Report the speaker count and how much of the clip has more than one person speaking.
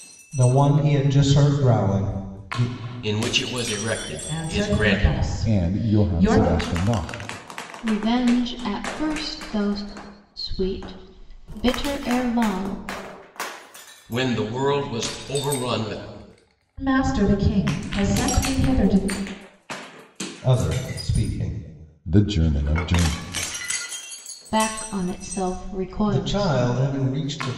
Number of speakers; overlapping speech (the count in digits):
5, about 9%